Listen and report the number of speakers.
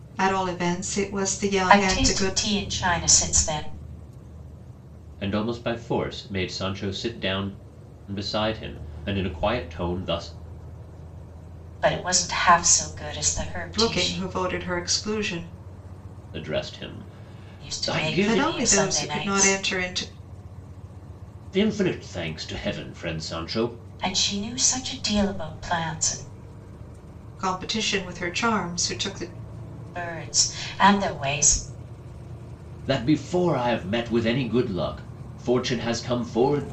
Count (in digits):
3